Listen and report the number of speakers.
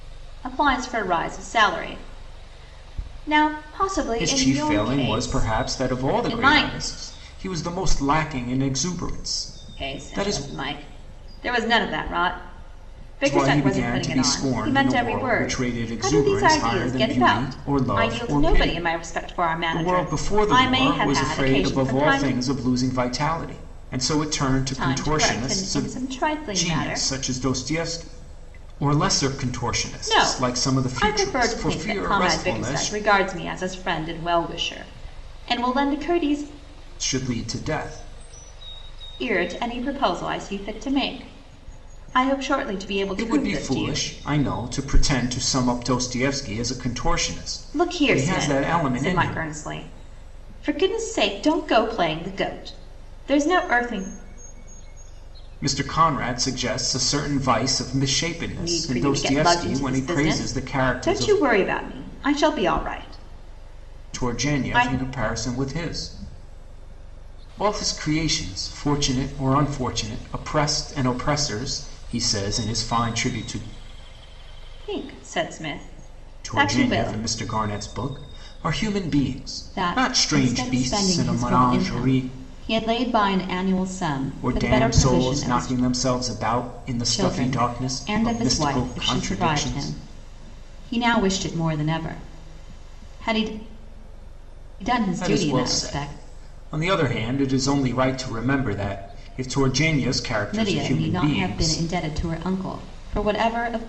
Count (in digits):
2